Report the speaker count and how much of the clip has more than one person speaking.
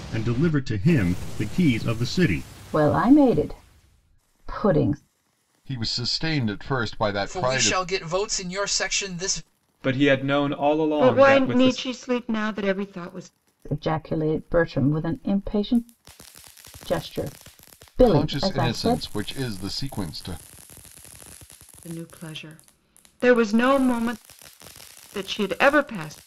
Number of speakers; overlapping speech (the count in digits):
6, about 10%